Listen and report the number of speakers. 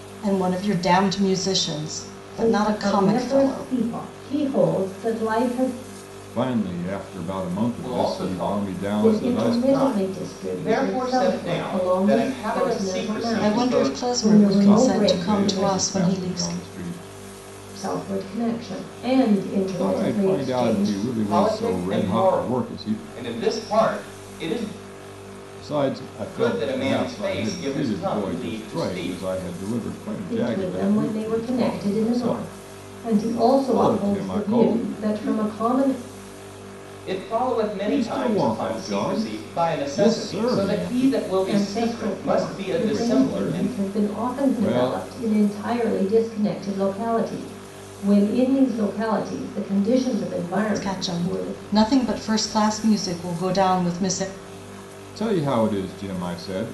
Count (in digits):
4